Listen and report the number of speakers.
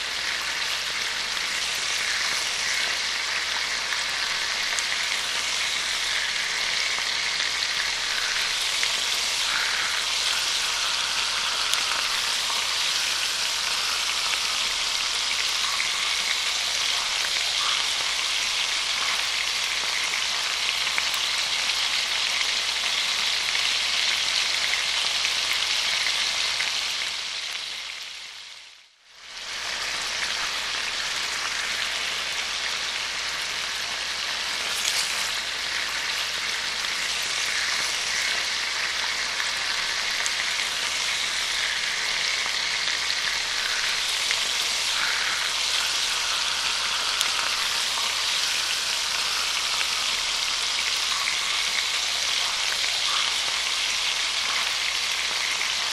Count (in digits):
0